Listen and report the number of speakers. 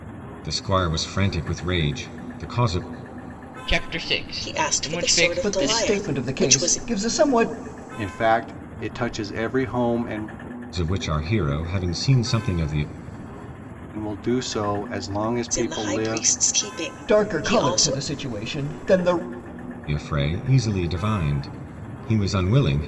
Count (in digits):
5